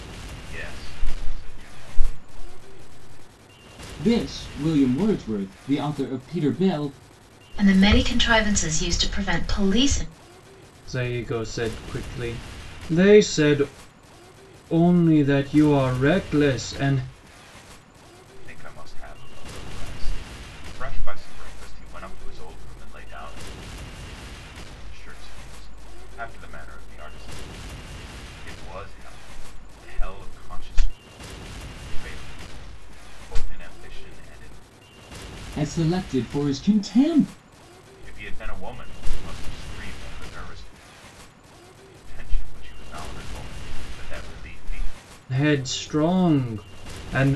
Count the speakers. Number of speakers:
4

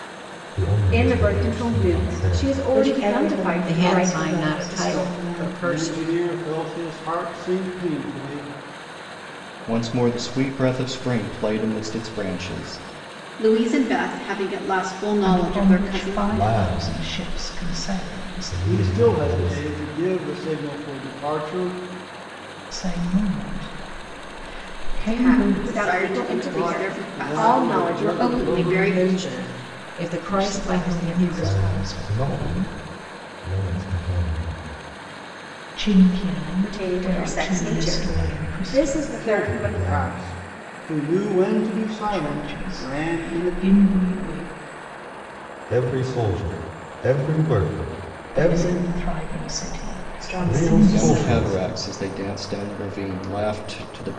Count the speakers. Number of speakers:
8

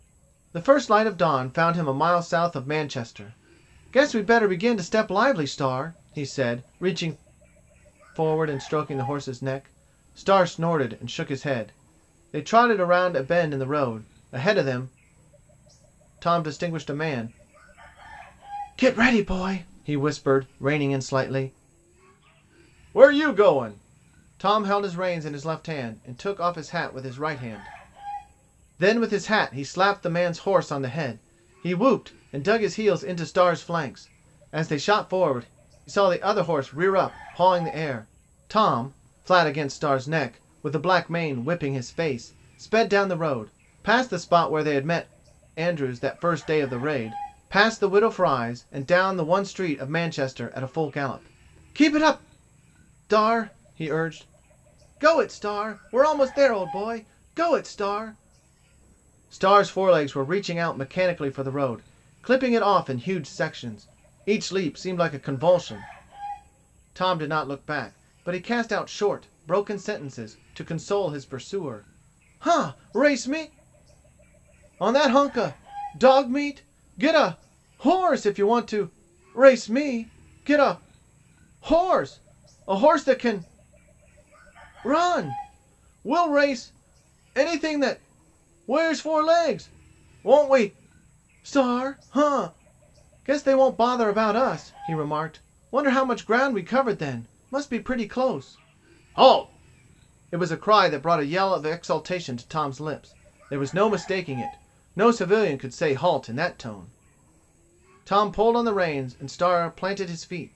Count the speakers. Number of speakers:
1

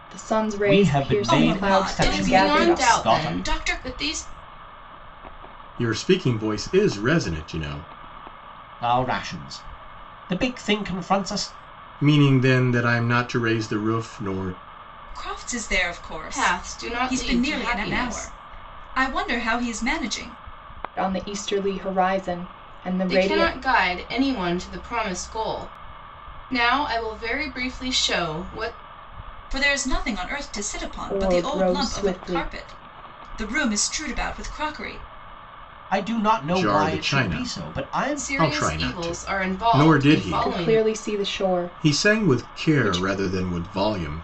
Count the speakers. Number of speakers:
5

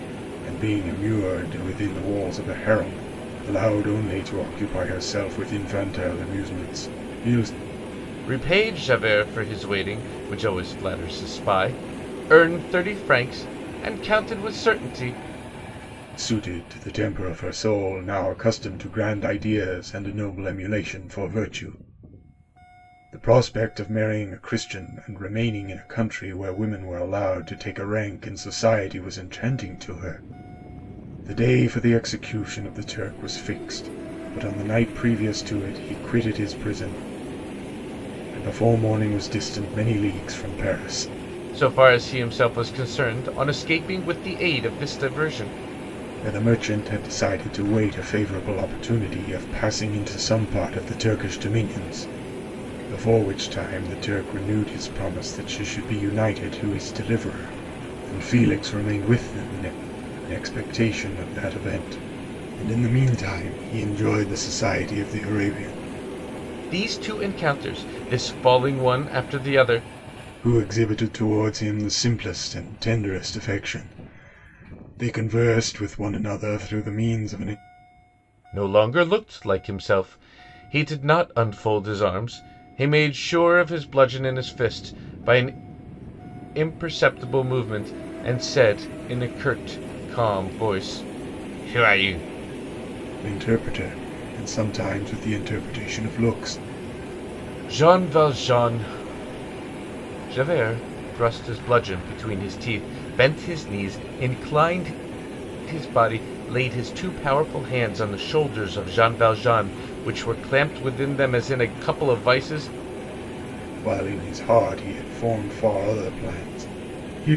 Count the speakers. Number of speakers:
2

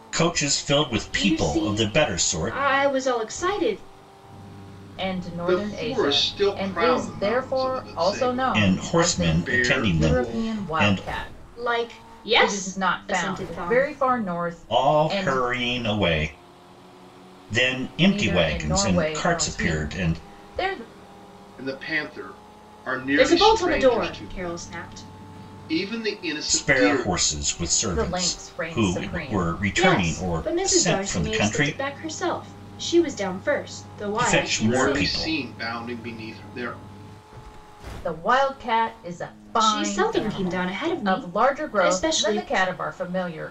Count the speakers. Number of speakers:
4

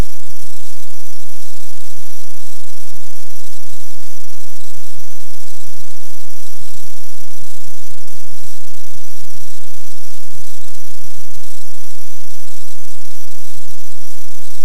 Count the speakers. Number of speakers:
0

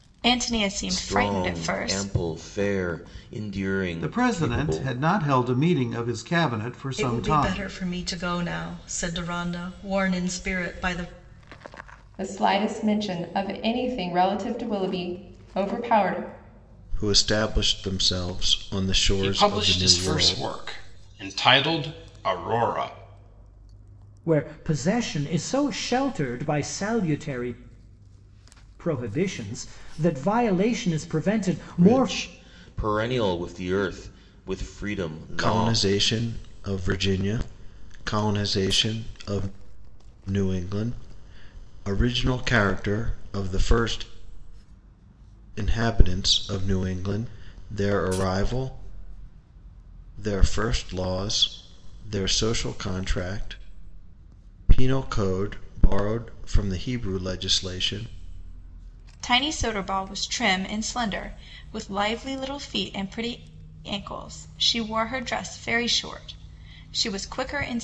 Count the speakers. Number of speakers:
8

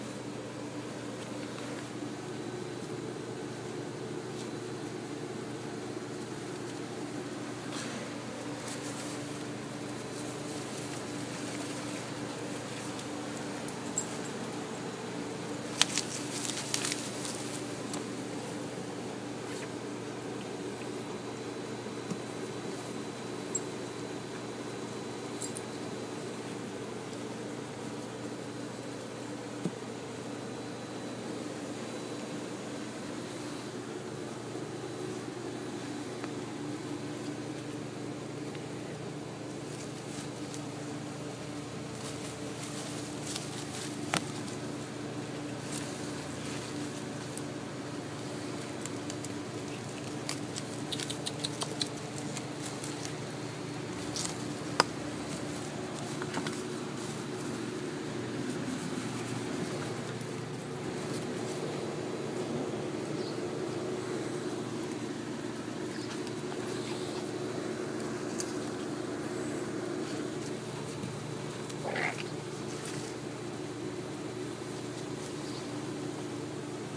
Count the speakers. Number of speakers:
0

